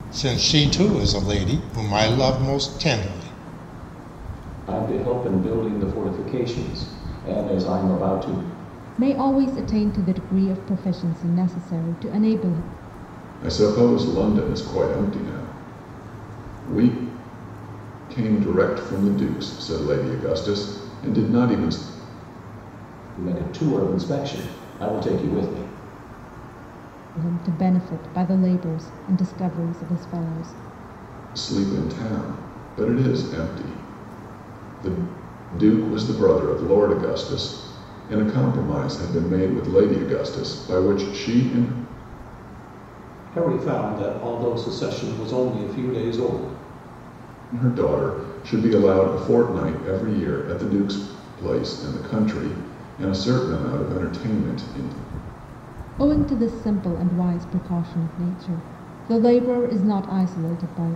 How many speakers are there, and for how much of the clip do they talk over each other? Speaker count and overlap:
4, no overlap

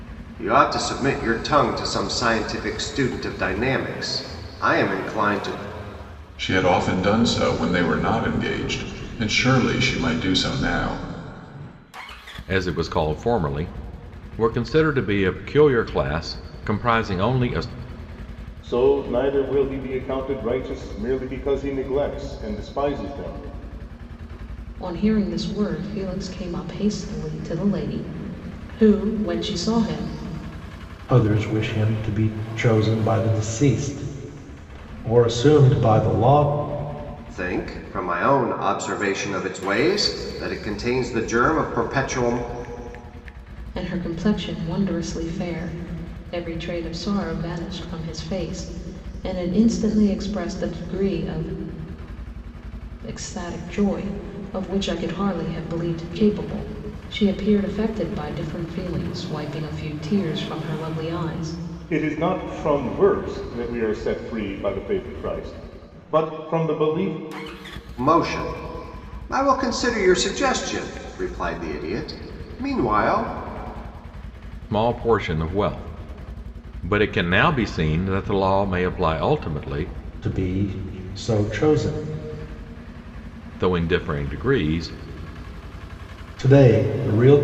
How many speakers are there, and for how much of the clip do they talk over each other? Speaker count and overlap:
6, no overlap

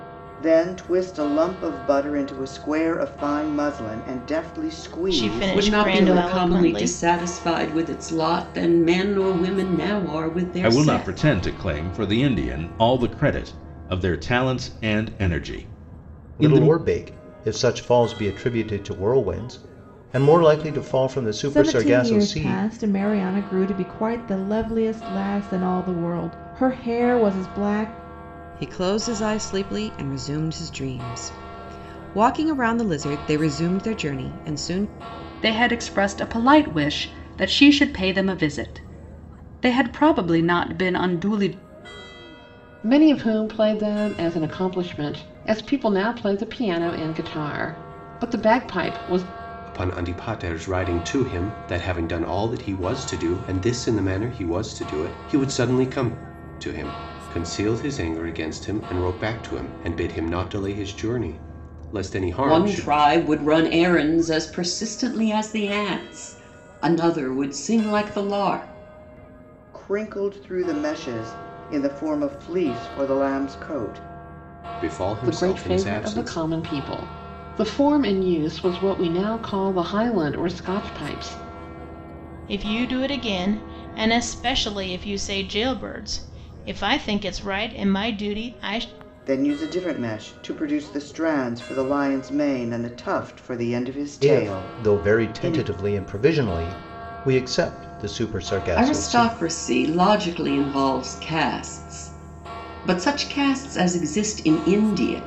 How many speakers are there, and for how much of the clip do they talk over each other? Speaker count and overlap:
10, about 8%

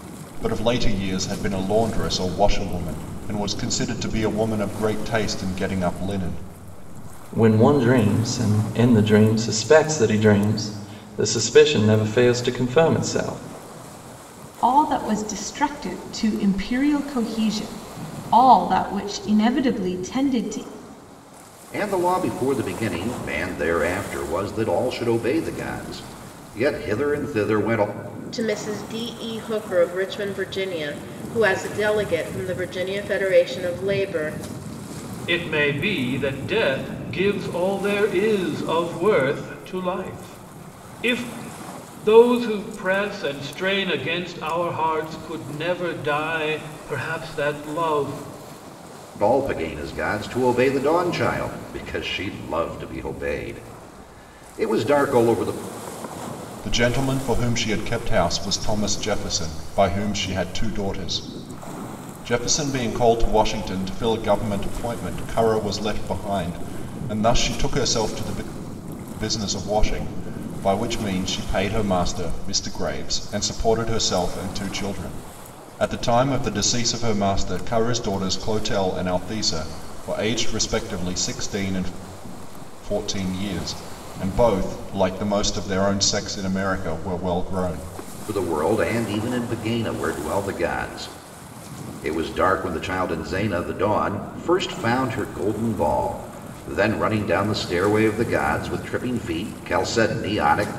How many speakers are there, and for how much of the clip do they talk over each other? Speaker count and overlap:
6, no overlap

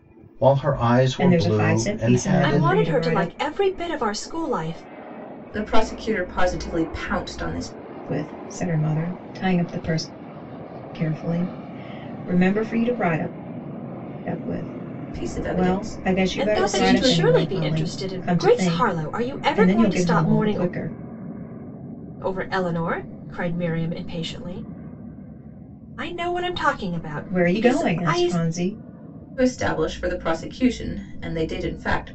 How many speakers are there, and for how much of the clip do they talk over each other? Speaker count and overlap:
4, about 26%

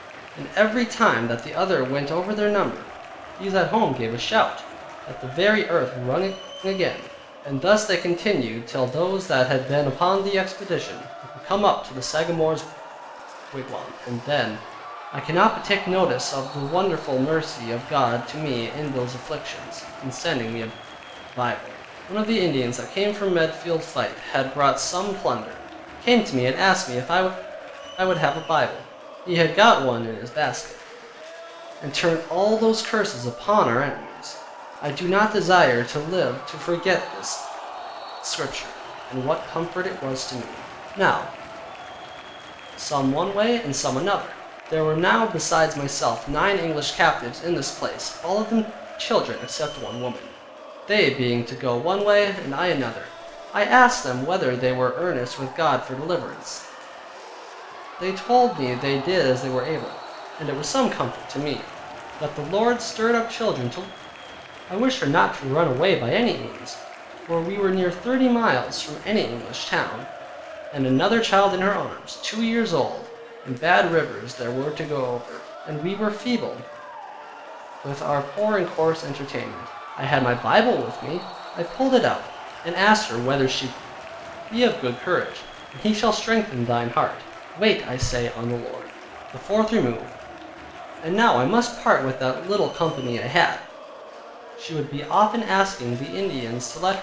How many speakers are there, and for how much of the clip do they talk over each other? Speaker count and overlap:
1, no overlap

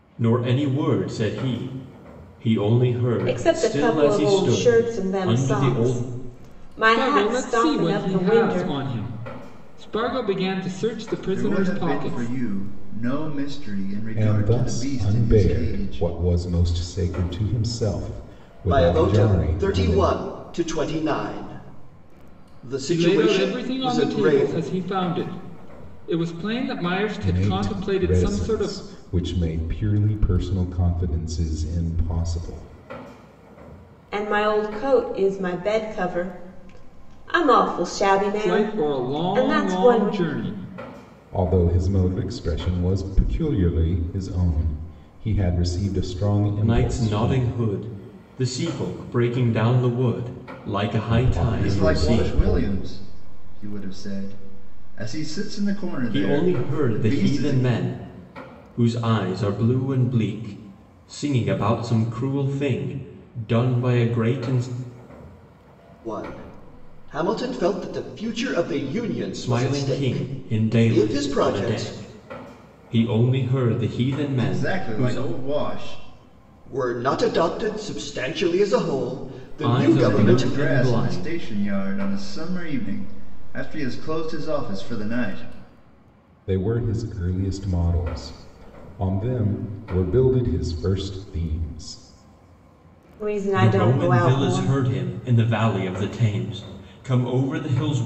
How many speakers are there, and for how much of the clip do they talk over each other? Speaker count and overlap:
6, about 26%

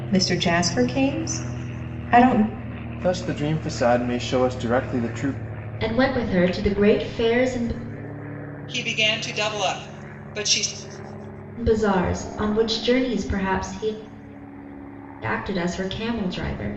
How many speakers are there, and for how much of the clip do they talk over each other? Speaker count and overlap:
4, no overlap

